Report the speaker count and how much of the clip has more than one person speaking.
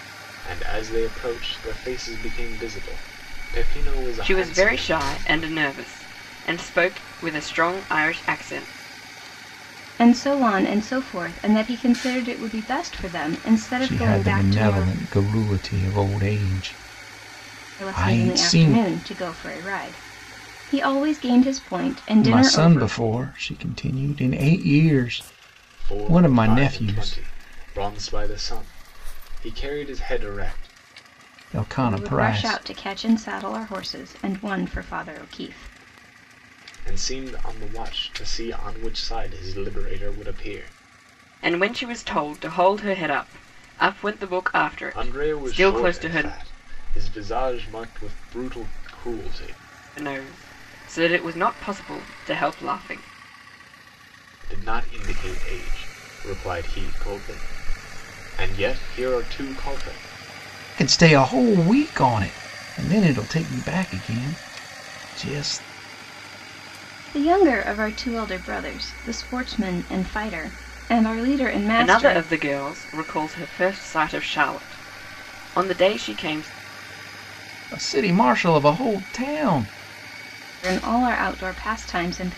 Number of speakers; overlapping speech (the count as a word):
four, about 10%